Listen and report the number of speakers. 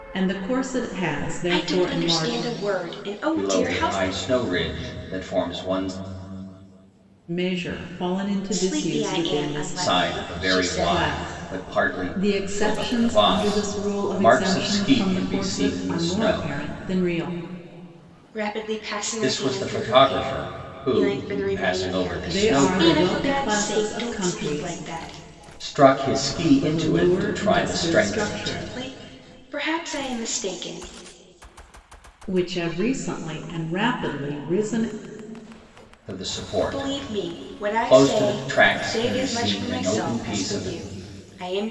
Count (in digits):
3